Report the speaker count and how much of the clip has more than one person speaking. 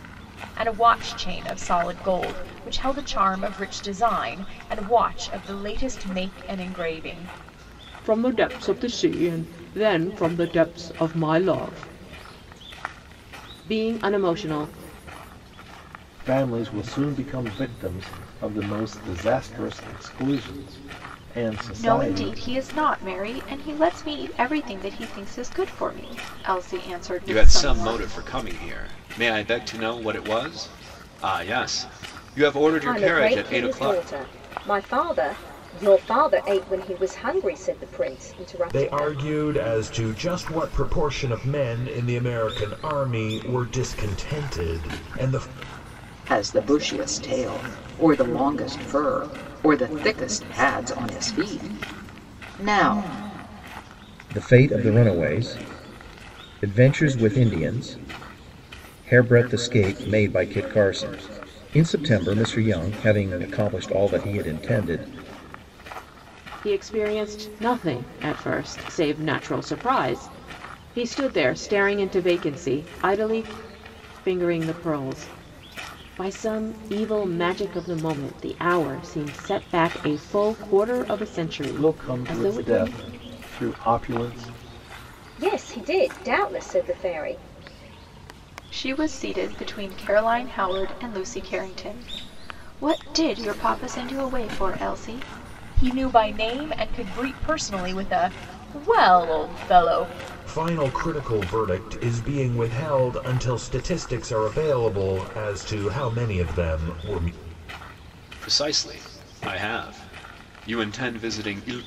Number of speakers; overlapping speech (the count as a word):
nine, about 4%